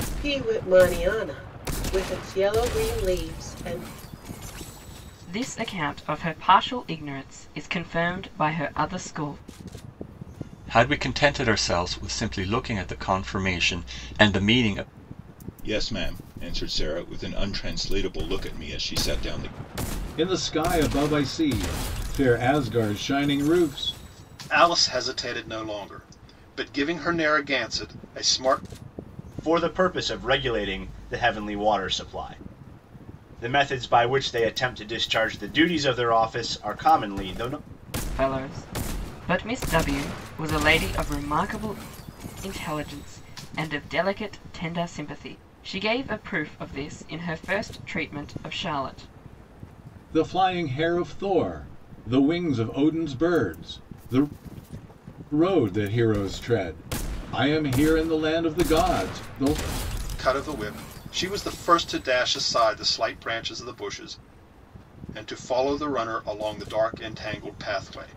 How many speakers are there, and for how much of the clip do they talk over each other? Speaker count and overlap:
seven, no overlap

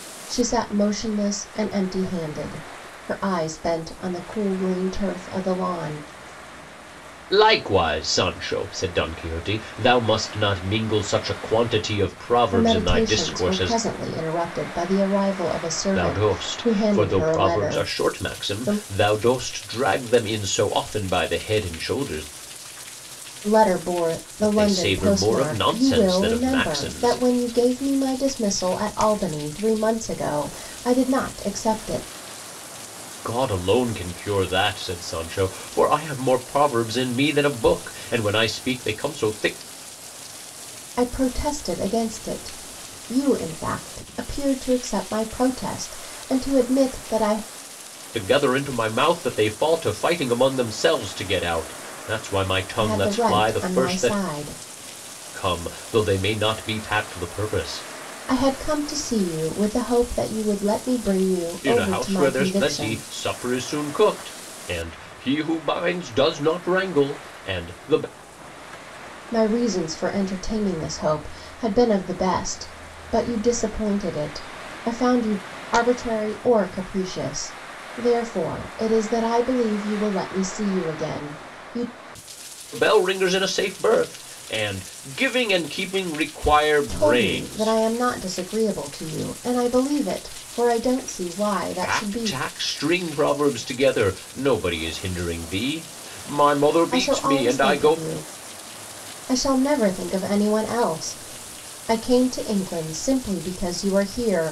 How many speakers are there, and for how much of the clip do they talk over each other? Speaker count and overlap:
two, about 12%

